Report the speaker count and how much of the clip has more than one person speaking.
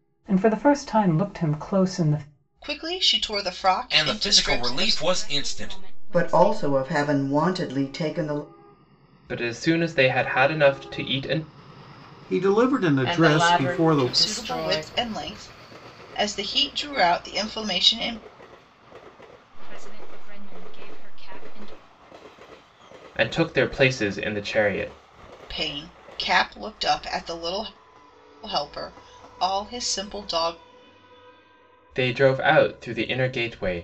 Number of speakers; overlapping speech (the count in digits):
8, about 13%